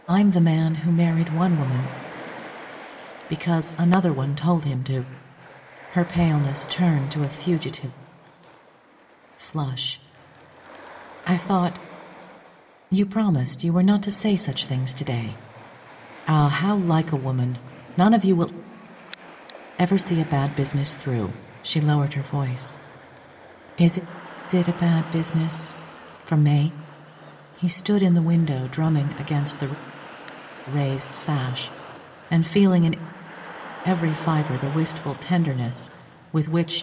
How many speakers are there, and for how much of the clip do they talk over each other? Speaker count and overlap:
1, no overlap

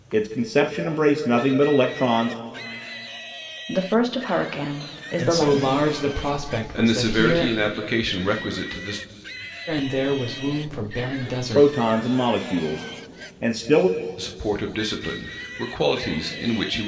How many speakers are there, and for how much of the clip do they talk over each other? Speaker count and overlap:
4, about 11%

